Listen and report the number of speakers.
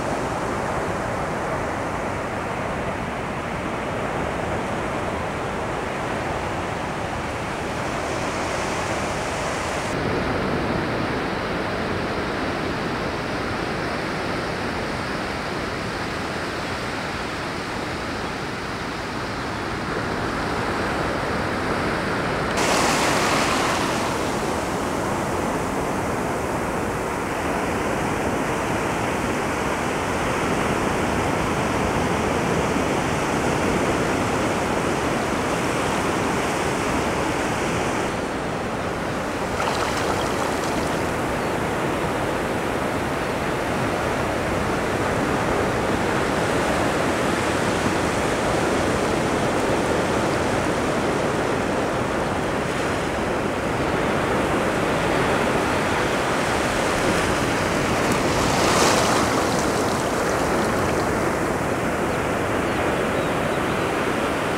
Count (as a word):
zero